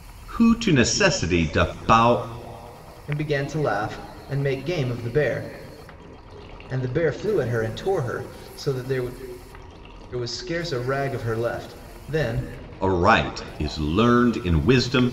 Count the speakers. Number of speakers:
2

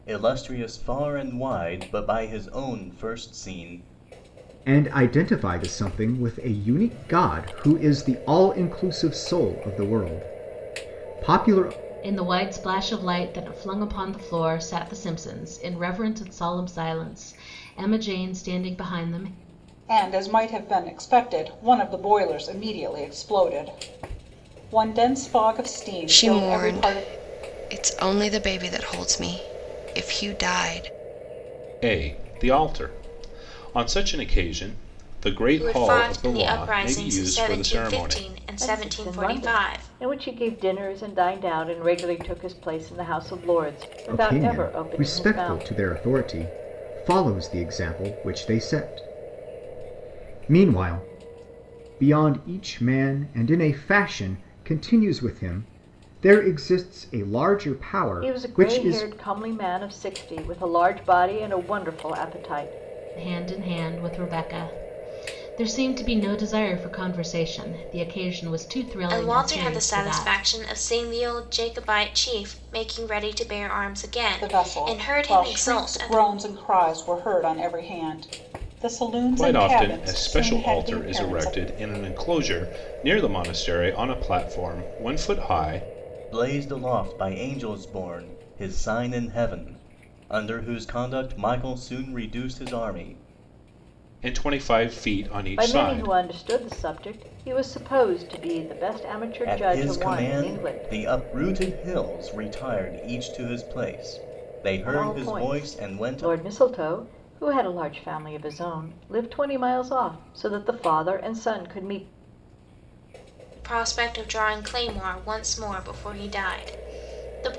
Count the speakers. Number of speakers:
8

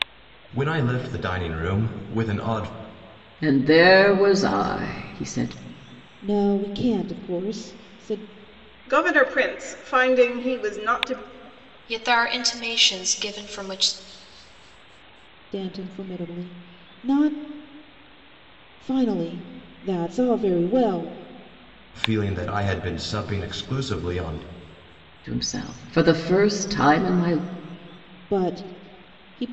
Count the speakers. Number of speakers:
5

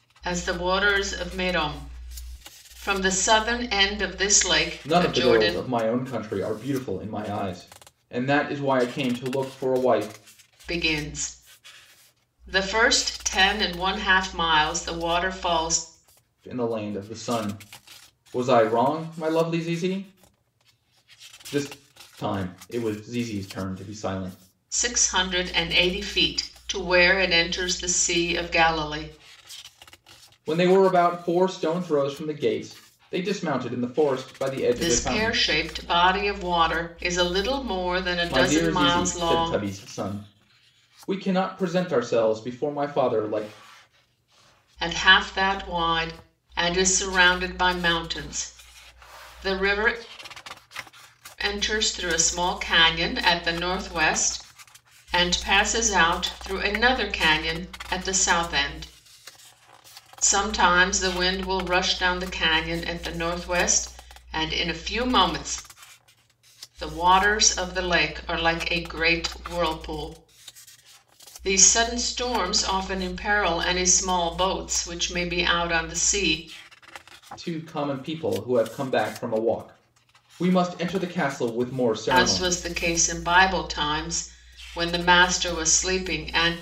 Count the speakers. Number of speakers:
2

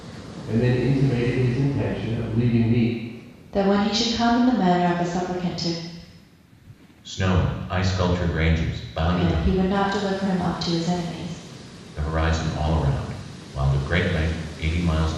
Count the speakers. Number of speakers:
3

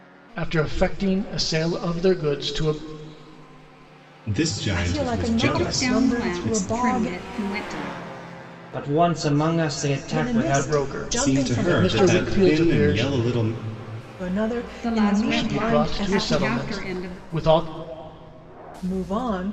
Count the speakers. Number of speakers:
5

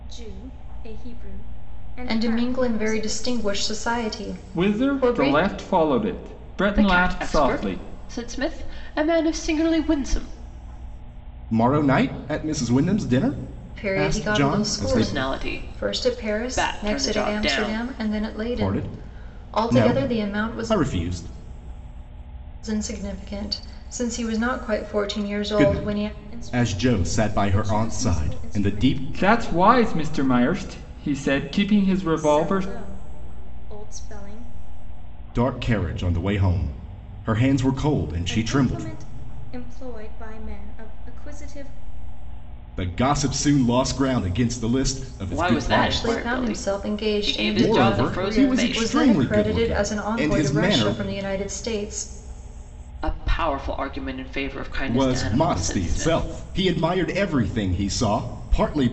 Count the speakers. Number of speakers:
5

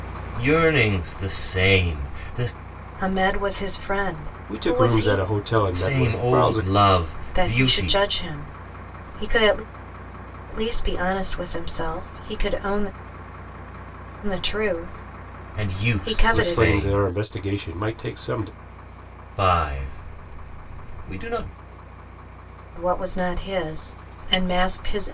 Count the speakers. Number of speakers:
3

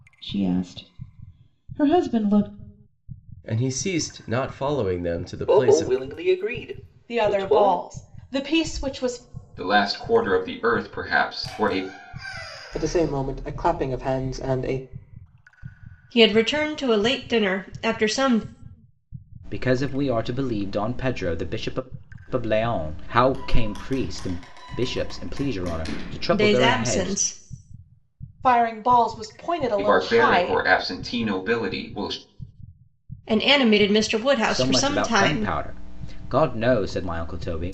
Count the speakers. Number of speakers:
8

